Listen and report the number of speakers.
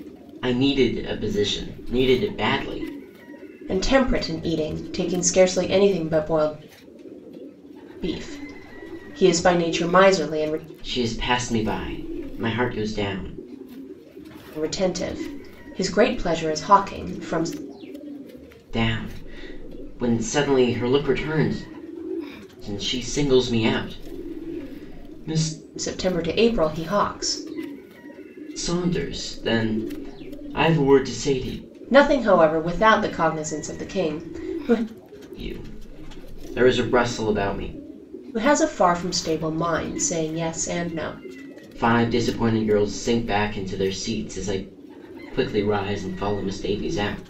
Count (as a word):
two